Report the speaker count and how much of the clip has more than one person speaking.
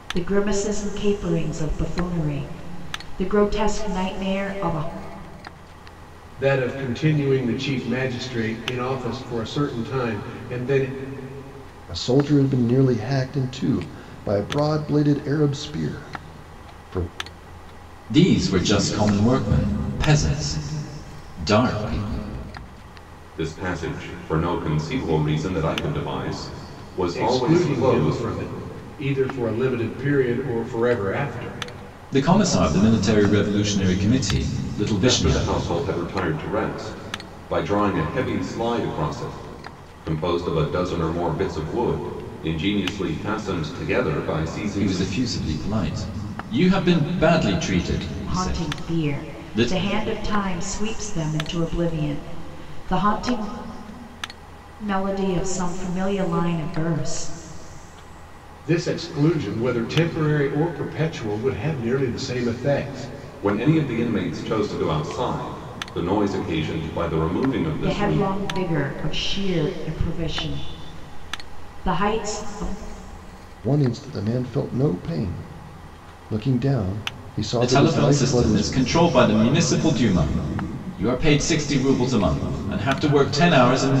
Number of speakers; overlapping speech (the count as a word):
five, about 6%